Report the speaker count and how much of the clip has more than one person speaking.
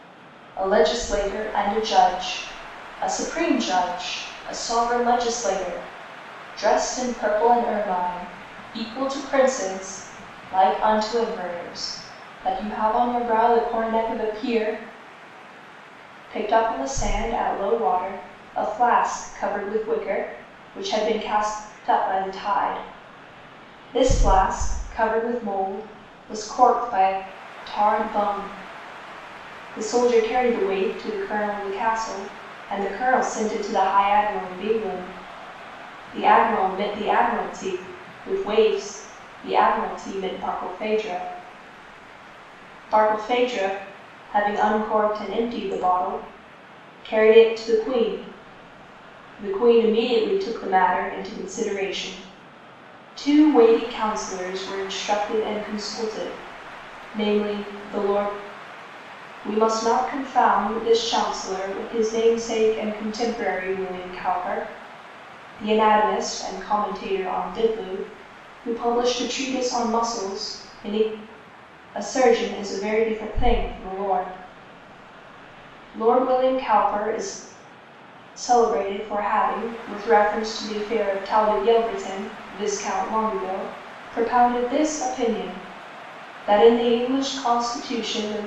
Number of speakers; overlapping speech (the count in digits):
1, no overlap